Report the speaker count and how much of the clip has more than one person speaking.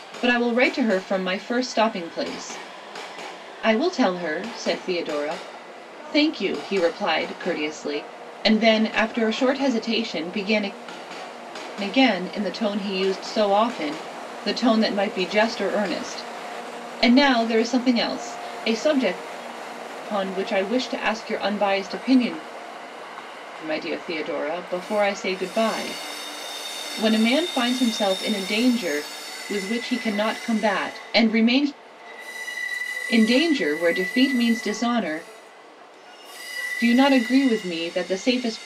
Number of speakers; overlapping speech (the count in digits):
1, no overlap